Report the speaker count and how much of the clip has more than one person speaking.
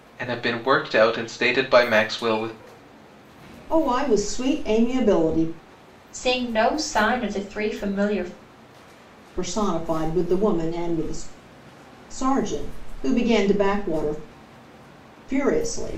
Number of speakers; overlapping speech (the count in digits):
3, no overlap